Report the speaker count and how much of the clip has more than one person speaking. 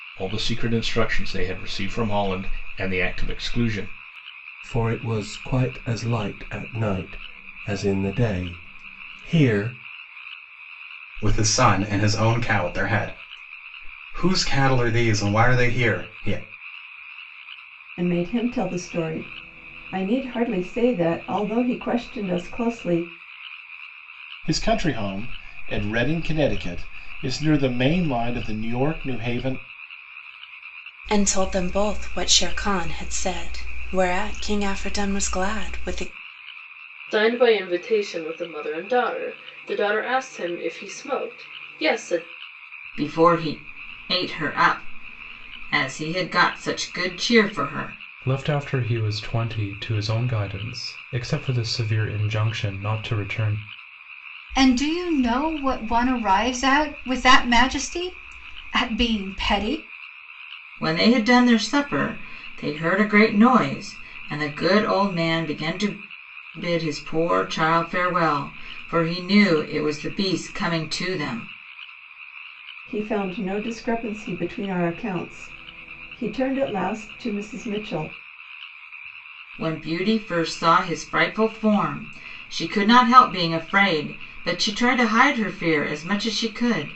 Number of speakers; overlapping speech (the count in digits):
10, no overlap